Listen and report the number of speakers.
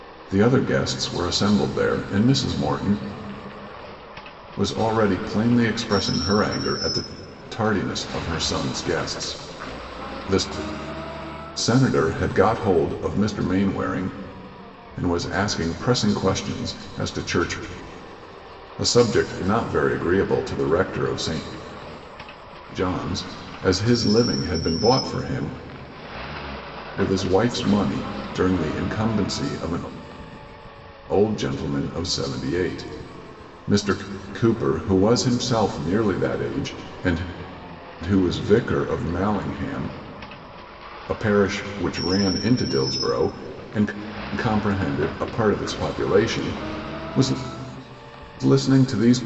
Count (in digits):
1